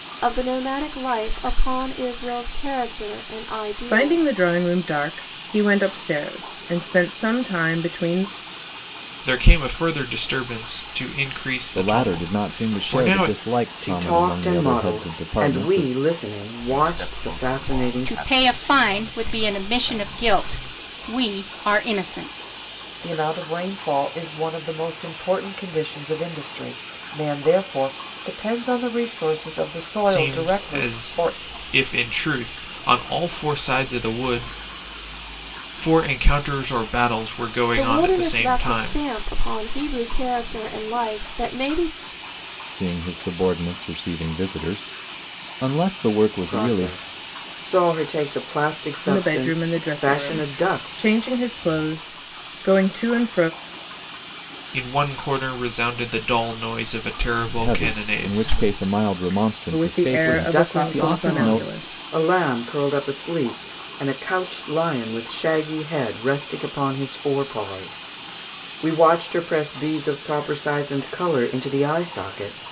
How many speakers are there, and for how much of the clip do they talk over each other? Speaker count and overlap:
8, about 24%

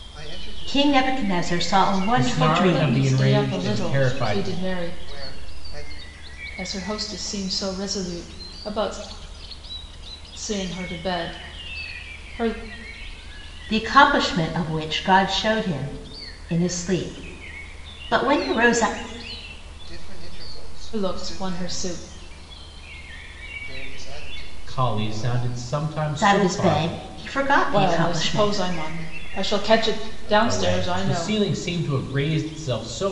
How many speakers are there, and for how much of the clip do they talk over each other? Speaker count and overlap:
4, about 32%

